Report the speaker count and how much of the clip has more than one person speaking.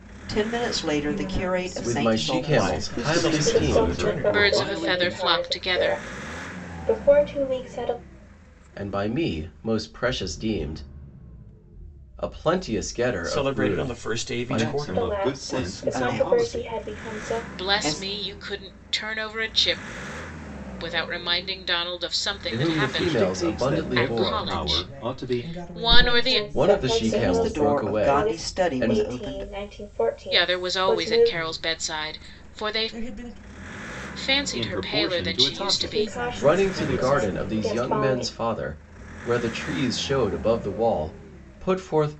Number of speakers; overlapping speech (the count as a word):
seven, about 55%